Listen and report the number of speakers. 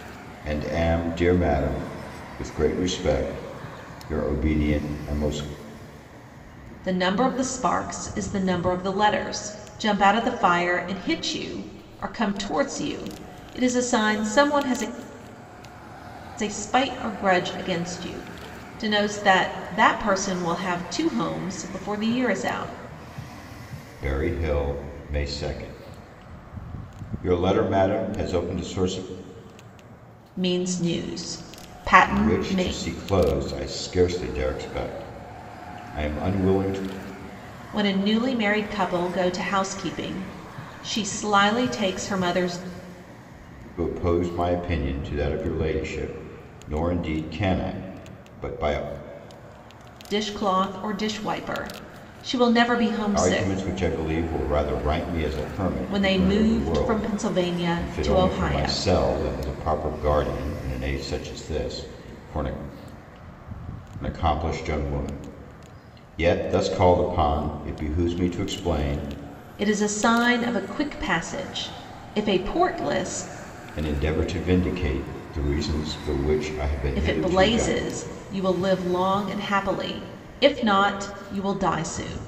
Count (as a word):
two